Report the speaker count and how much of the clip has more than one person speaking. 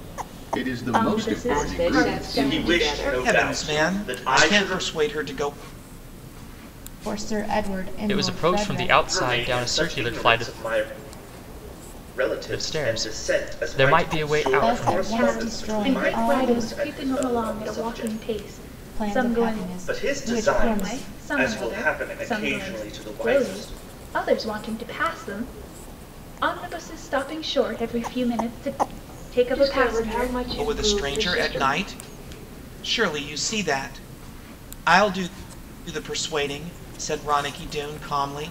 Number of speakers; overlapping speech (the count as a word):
seven, about 48%